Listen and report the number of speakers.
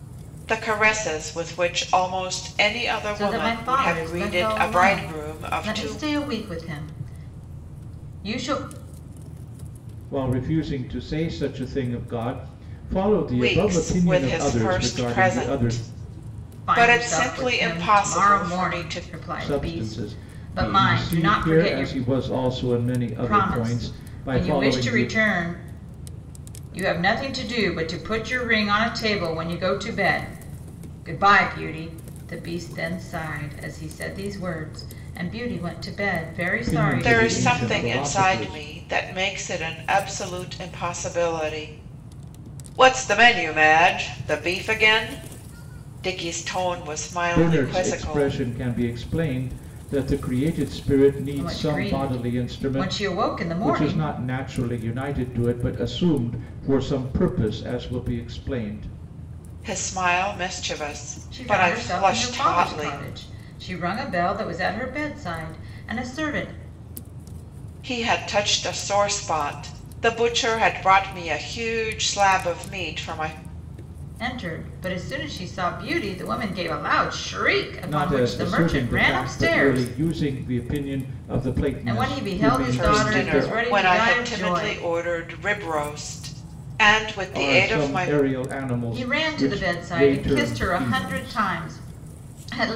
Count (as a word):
three